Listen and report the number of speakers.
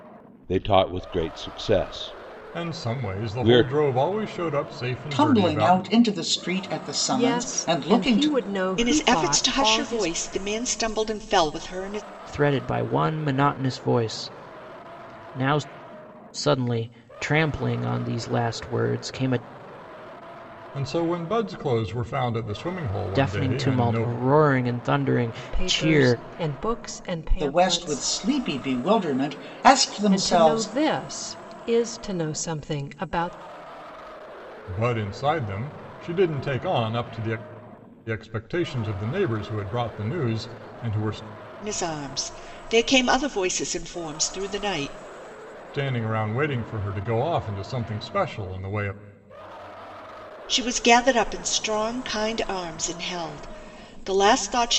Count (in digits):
6